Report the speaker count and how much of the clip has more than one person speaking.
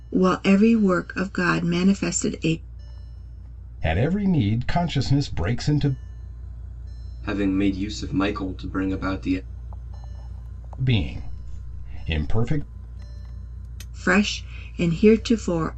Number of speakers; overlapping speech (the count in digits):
3, no overlap